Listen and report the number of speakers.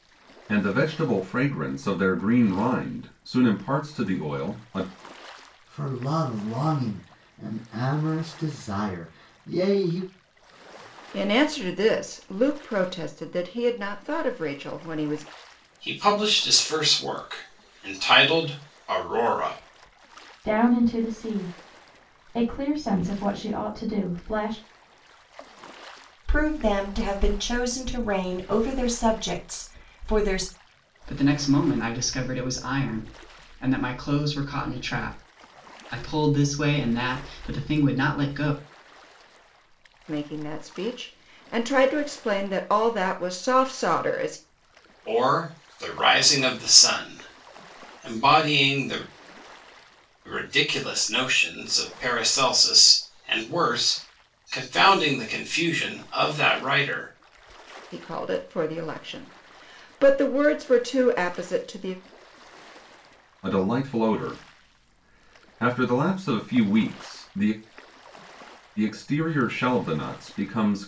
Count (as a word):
seven